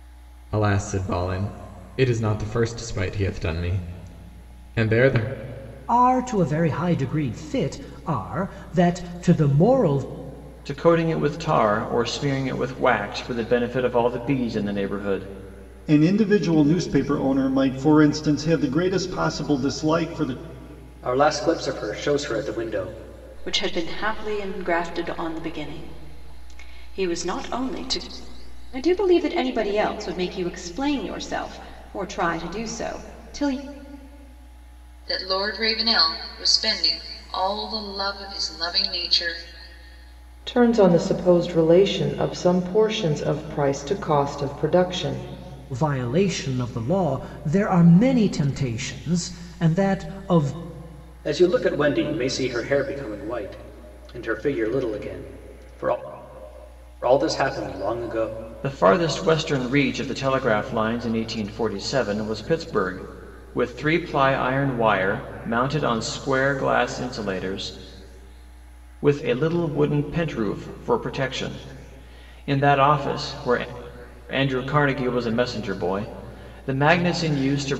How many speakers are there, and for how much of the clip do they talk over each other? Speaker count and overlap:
9, no overlap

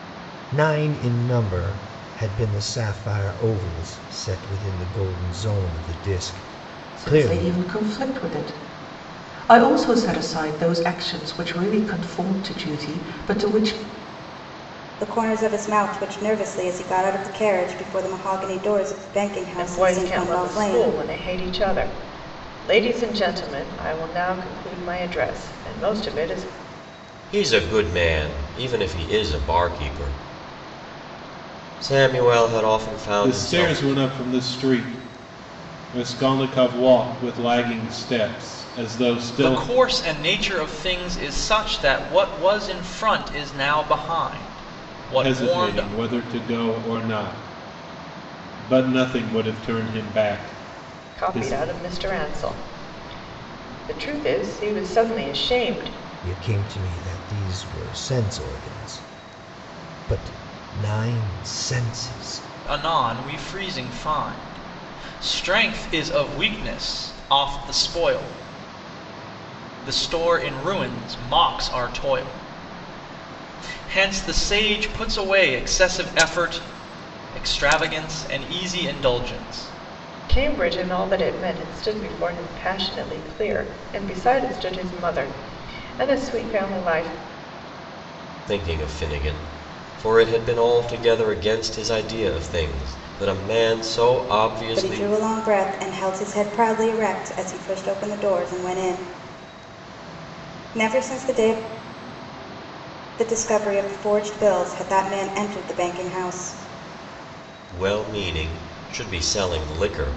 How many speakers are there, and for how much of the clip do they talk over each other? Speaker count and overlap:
7, about 4%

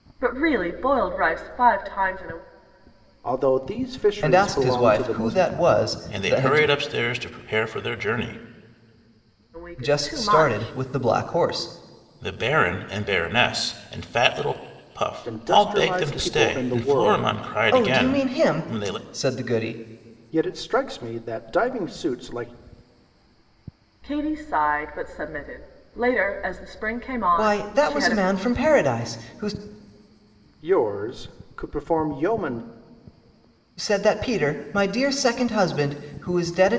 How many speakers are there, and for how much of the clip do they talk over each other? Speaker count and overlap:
4, about 20%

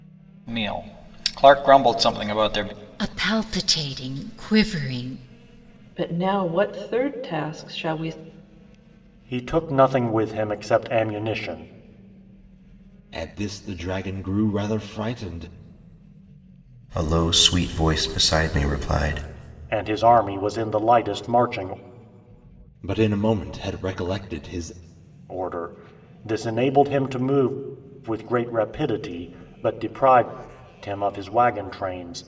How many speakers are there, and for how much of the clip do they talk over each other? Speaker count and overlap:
6, no overlap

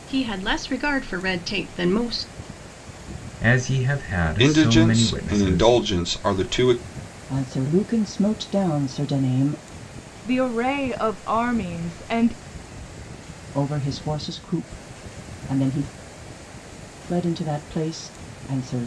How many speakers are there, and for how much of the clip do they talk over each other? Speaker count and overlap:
5, about 7%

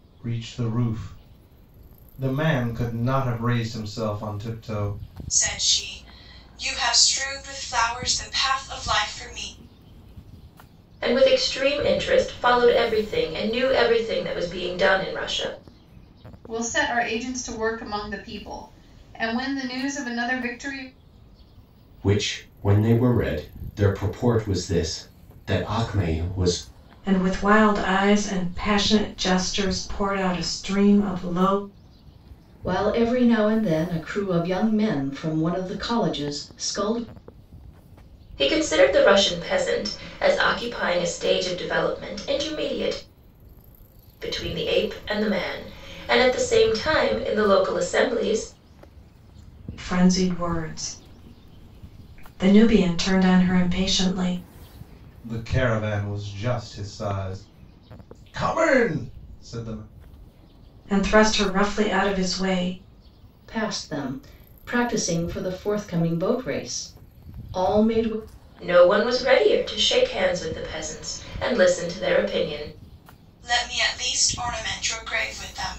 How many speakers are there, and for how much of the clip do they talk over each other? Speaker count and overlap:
7, no overlap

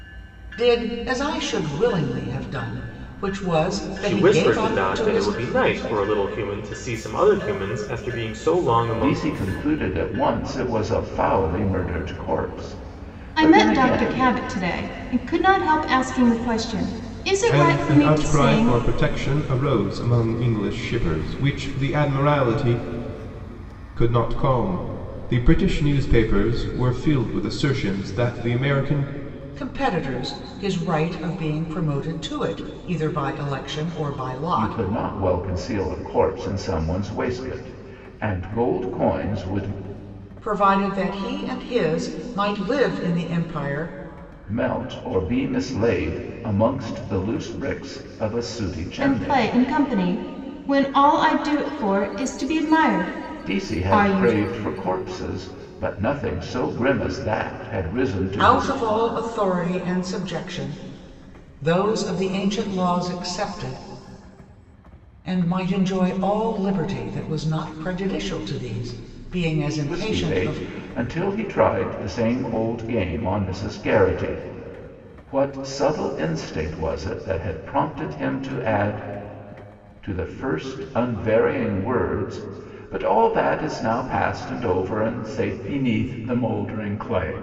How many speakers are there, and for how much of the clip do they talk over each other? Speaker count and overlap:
5, about 8%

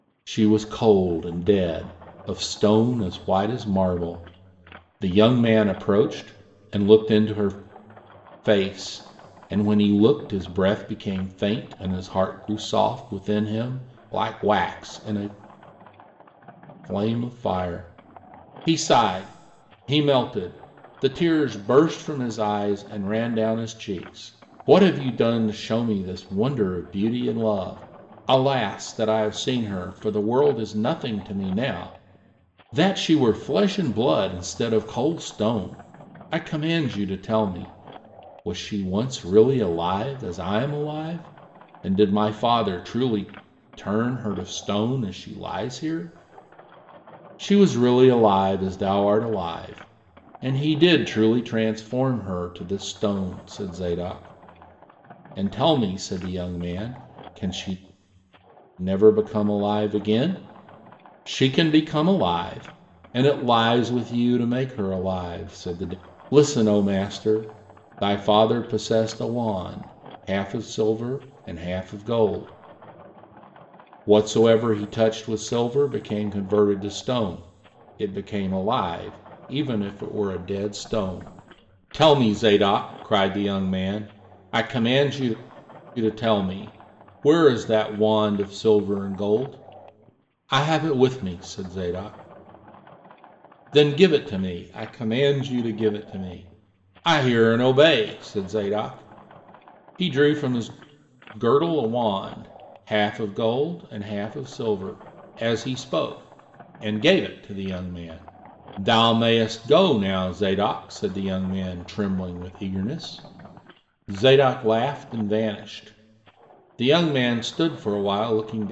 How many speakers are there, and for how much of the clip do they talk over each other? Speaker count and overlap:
1, no overlap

